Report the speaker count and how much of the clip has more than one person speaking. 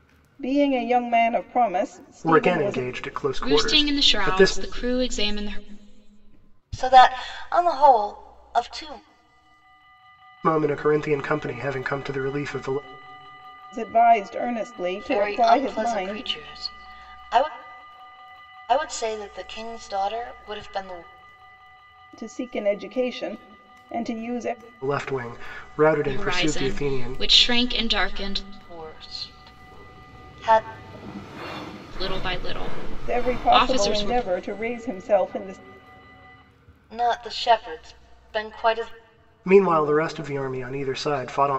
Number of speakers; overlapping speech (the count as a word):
four, about 13%